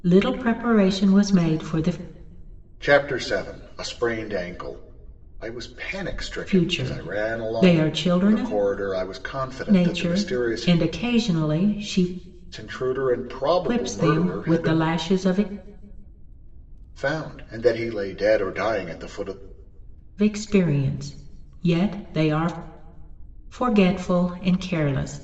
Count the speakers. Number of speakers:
2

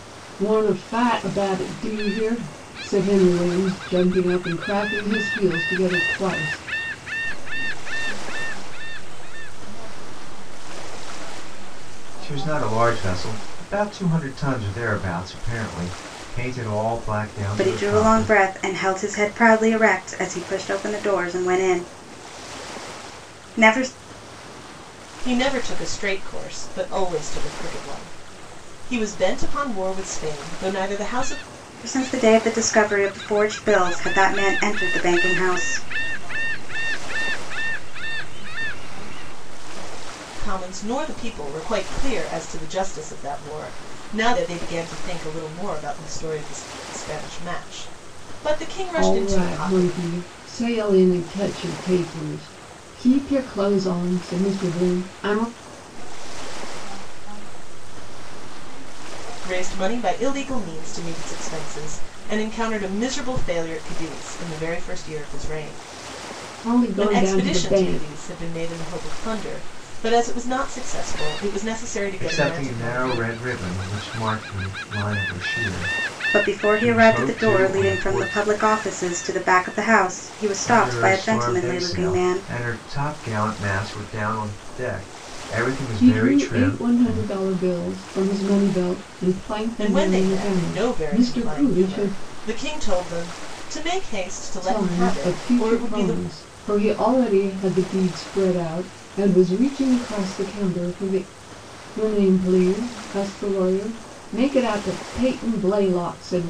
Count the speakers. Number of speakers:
5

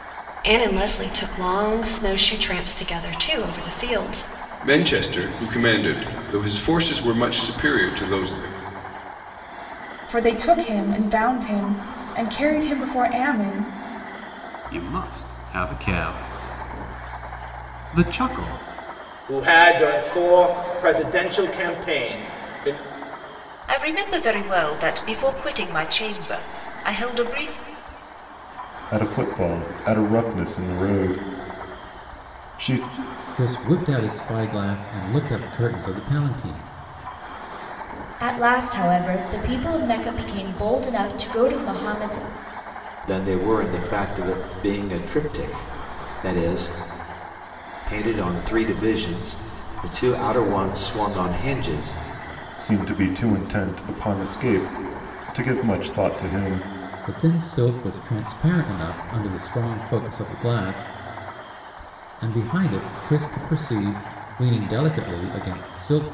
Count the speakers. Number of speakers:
10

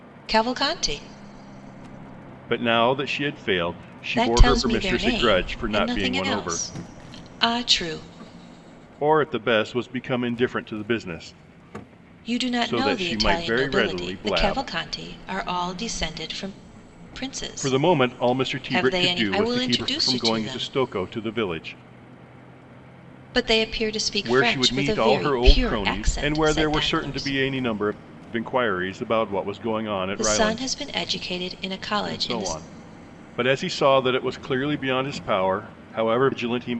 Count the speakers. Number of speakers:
2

